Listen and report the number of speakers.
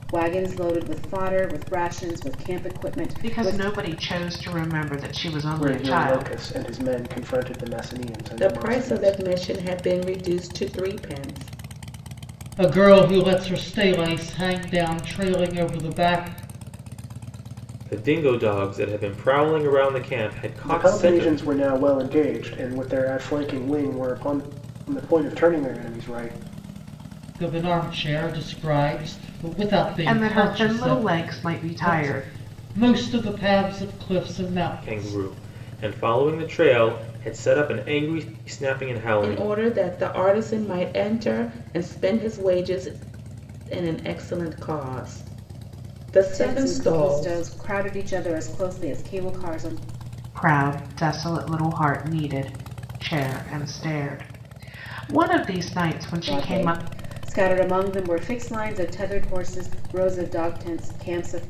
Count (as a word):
six